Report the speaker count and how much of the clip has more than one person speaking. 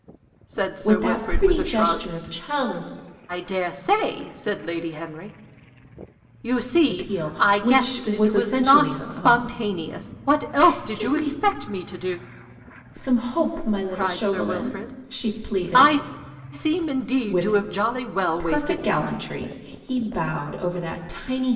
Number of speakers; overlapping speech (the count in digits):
2, about 45%